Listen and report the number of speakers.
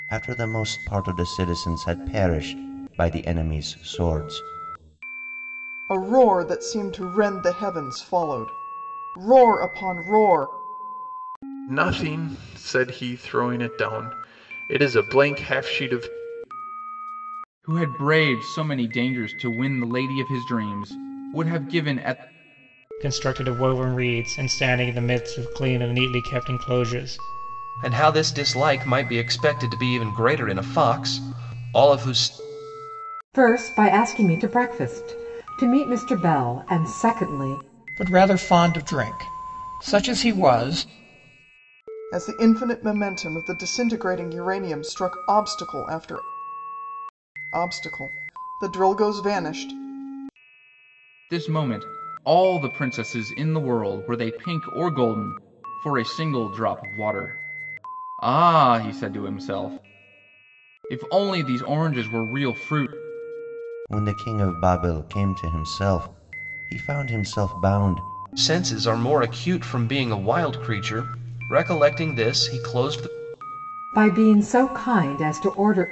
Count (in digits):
8